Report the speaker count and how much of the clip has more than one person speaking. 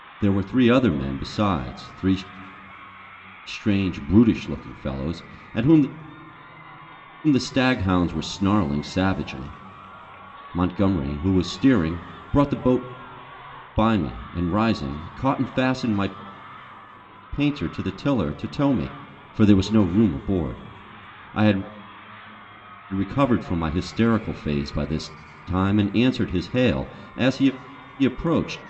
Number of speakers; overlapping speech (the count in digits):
1, no overlap